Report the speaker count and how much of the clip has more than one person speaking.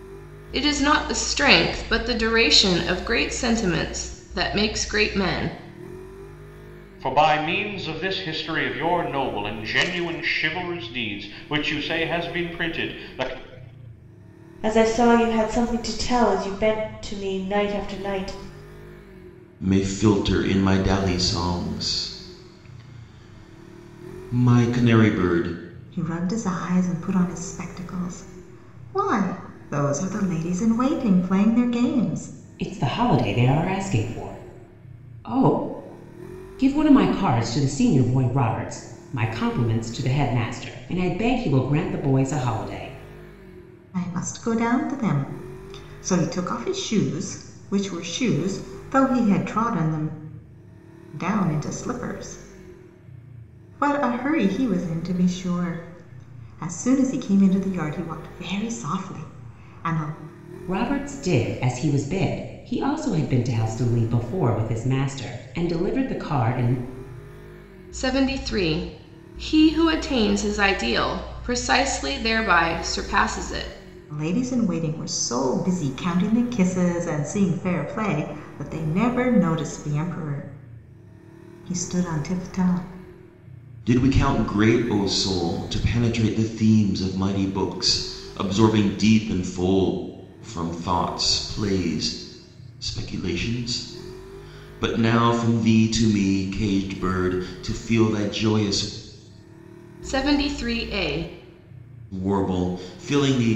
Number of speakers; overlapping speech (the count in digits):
6, no overlap